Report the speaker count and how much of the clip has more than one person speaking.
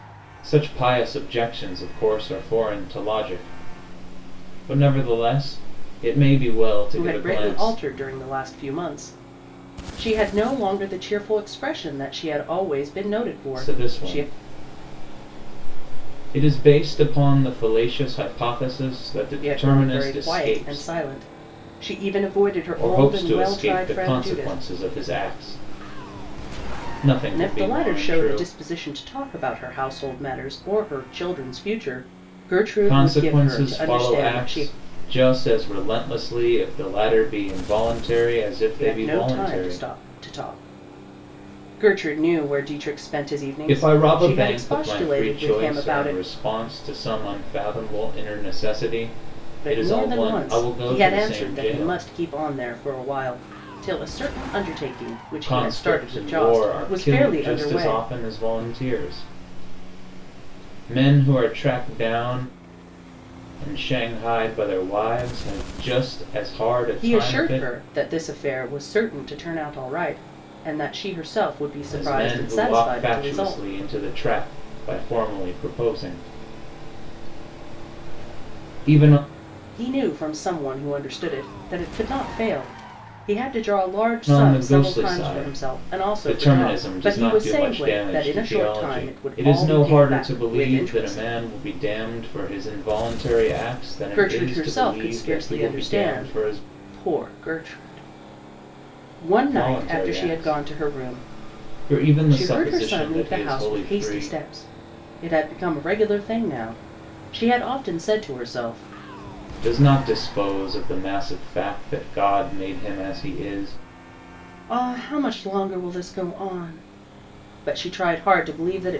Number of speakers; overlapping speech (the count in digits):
2, about 27%